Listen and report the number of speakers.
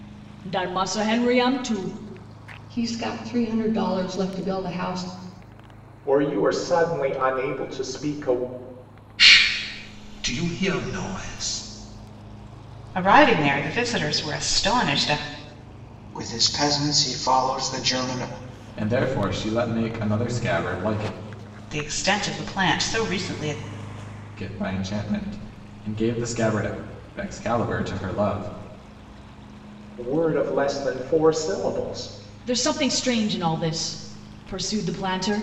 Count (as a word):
seven